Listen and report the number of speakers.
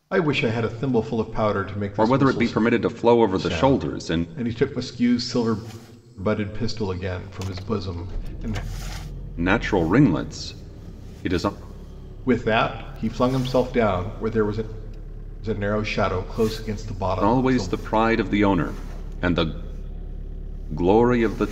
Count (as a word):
two